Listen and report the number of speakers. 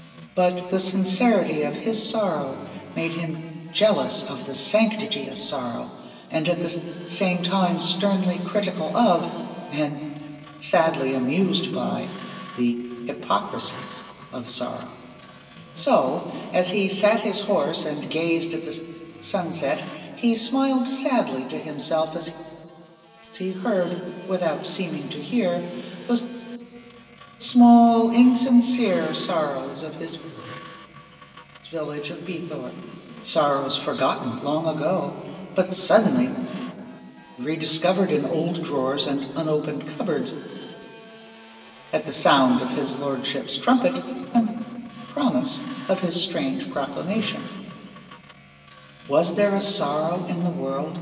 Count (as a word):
one